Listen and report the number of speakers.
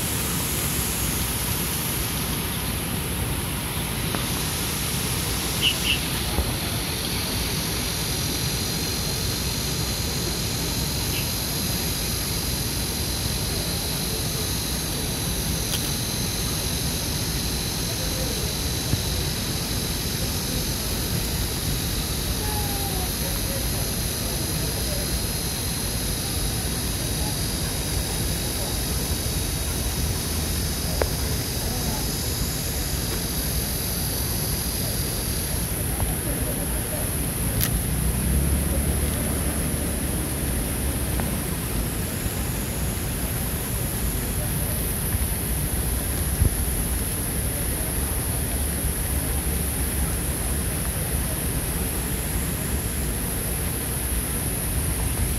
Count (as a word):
zero